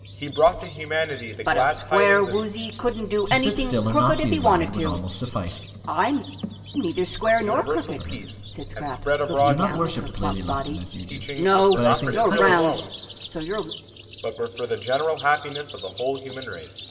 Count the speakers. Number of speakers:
3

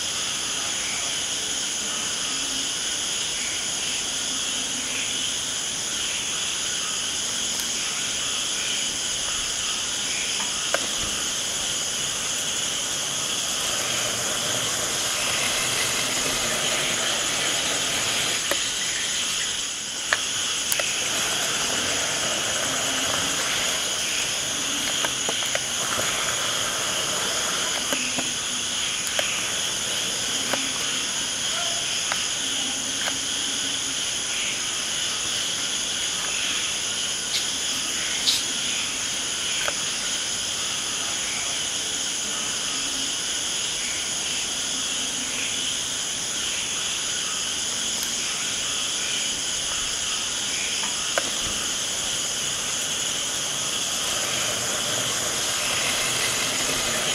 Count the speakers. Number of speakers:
0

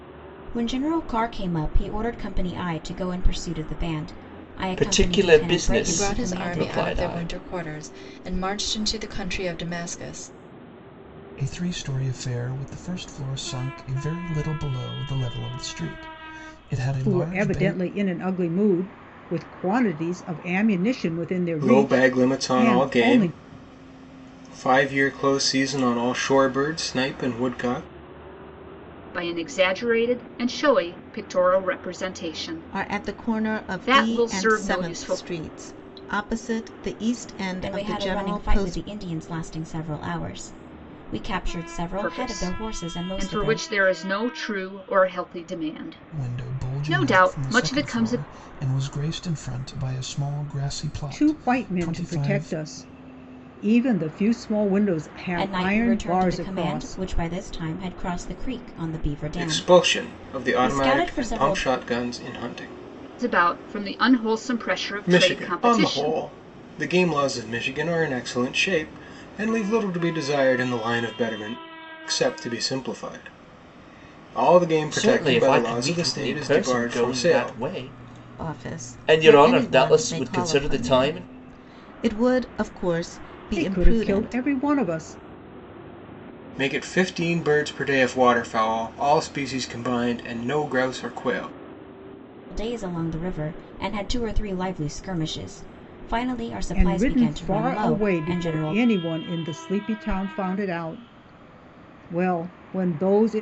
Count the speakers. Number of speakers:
8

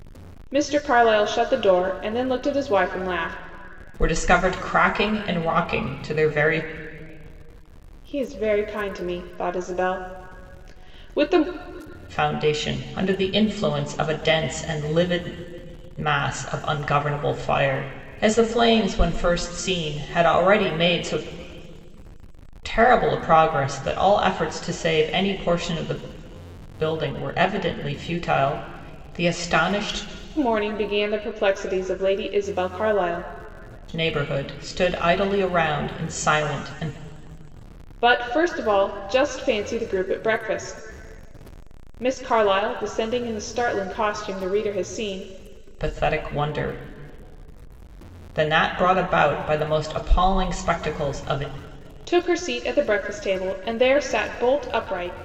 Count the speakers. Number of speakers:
2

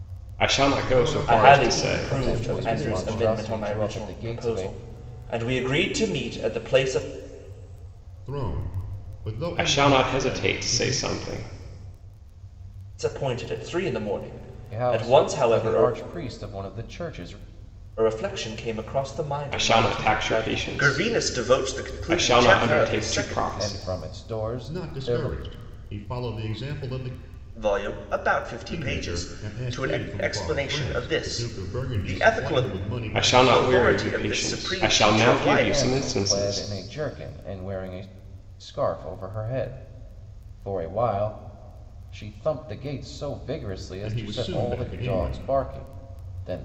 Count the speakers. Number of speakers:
4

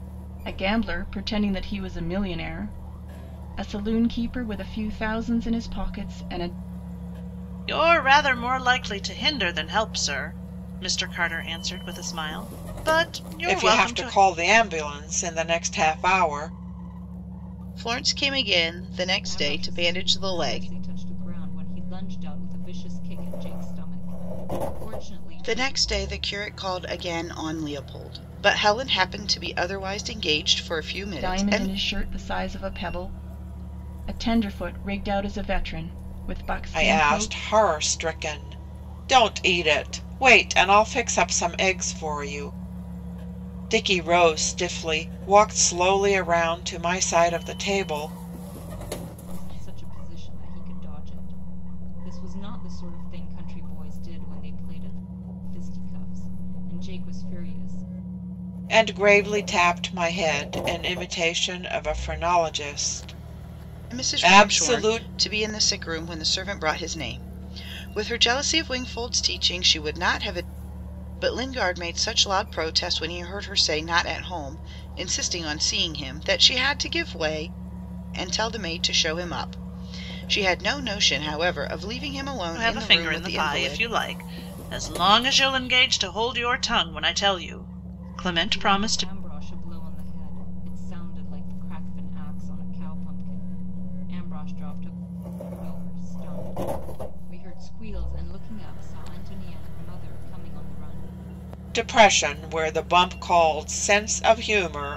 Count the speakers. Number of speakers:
5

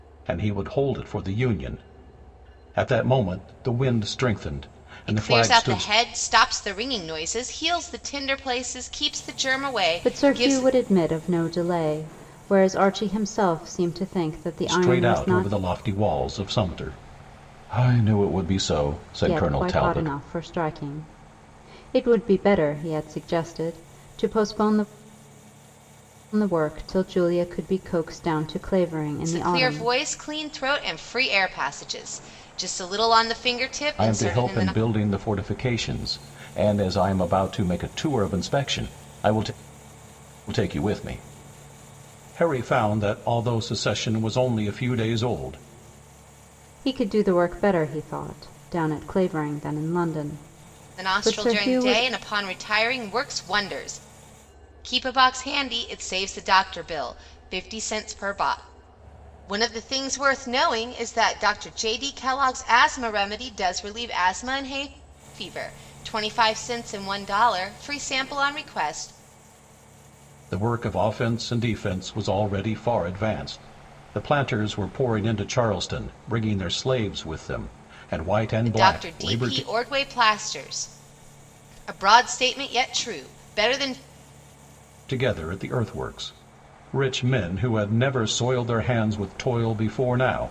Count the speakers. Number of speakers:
3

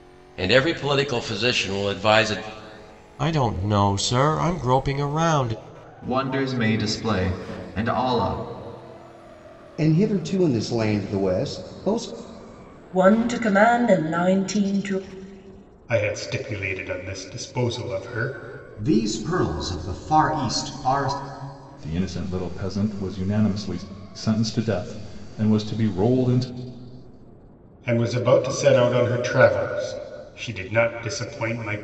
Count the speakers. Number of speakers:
8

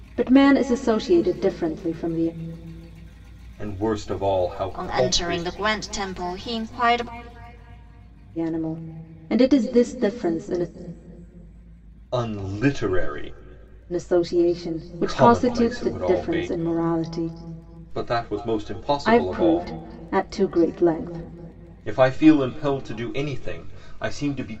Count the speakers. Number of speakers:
3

